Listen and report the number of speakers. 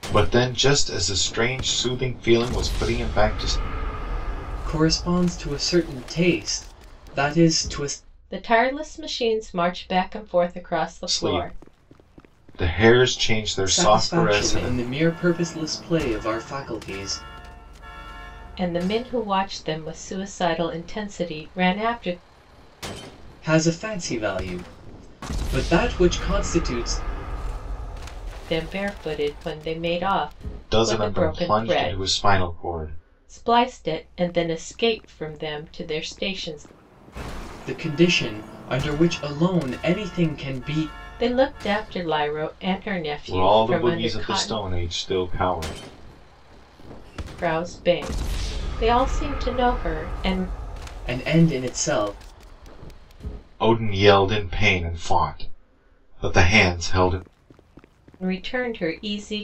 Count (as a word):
three